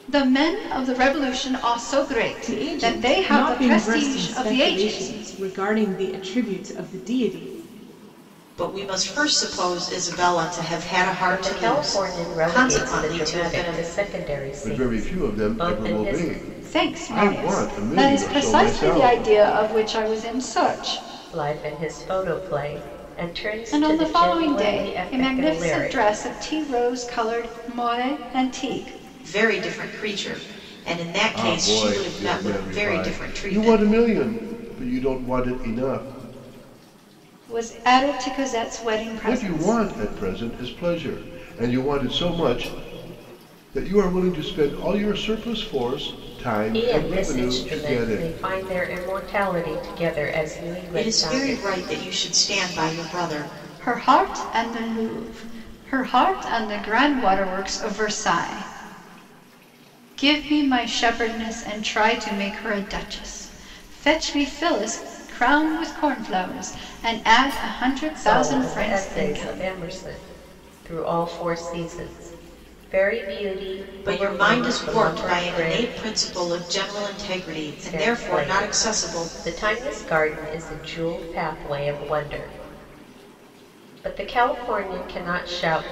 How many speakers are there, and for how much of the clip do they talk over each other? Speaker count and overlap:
five, about 27%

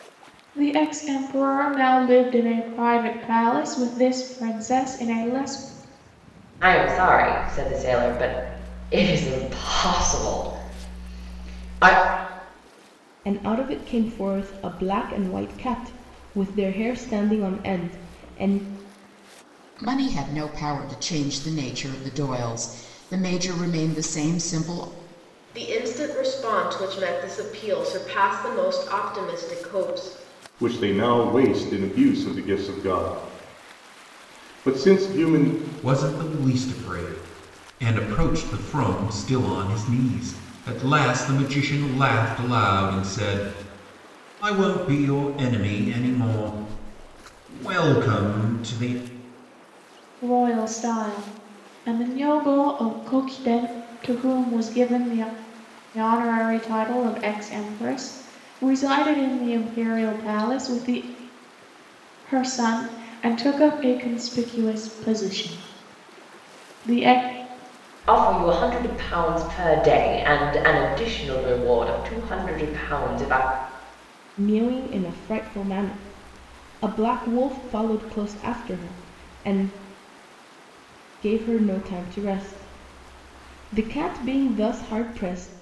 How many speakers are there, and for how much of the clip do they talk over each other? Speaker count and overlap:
seven, no overlap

